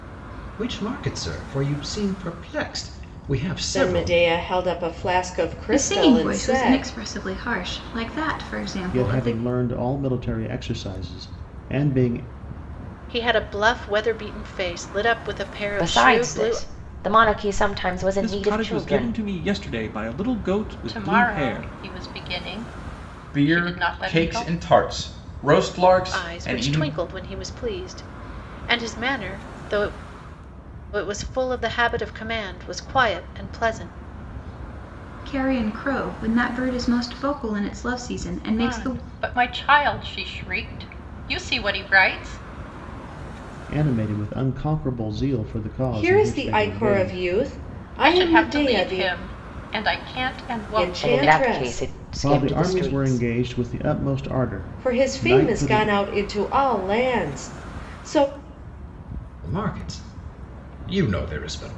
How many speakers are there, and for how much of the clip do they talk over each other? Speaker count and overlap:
9, about 22%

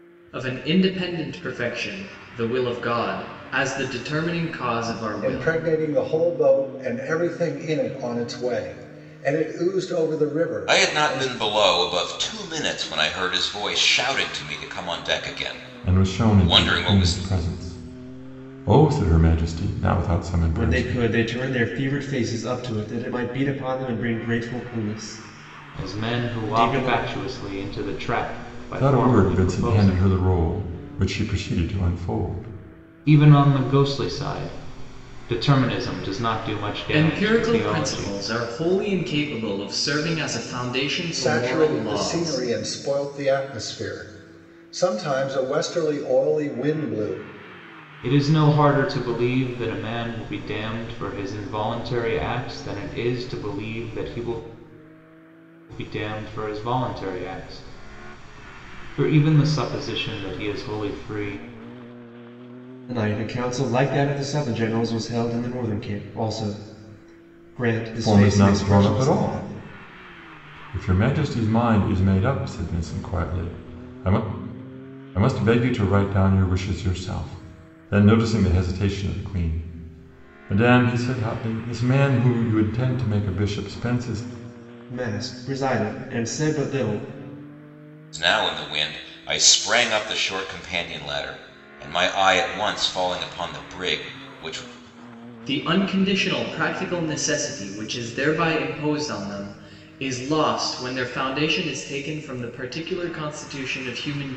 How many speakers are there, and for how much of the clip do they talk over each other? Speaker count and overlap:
6, about 9%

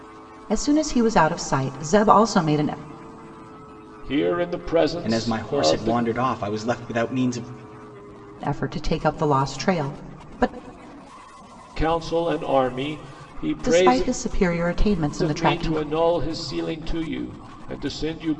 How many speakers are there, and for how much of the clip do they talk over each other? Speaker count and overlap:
3, about 12%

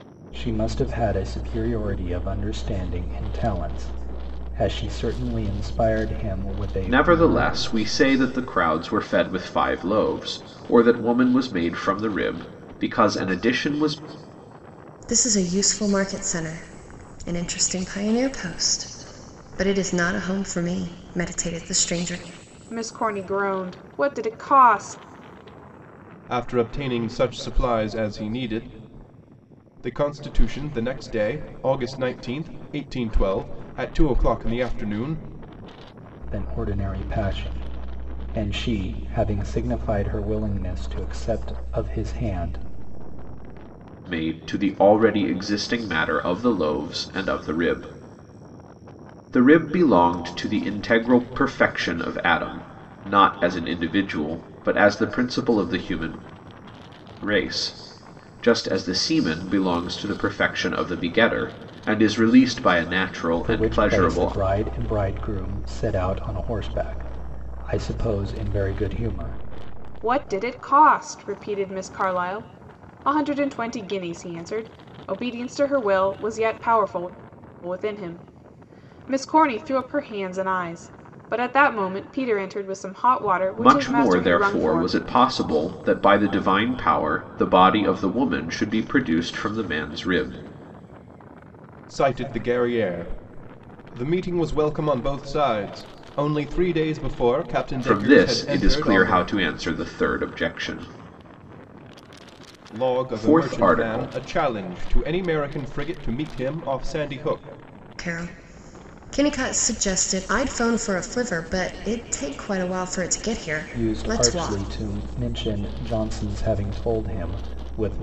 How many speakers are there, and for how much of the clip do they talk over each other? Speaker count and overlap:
5, about 6%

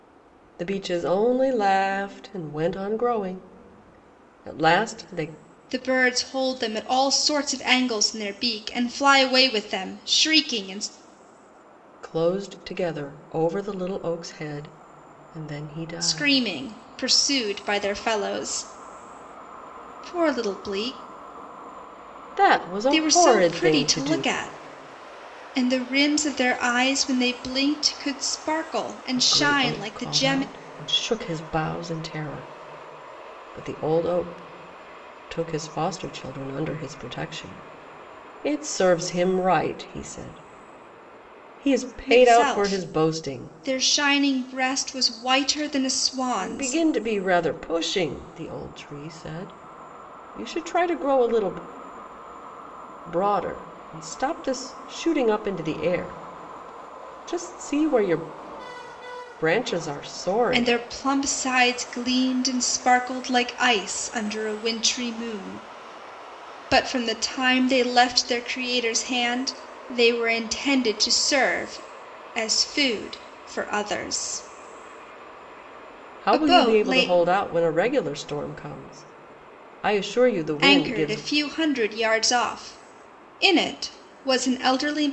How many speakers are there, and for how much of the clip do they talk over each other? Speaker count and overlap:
2, about 8%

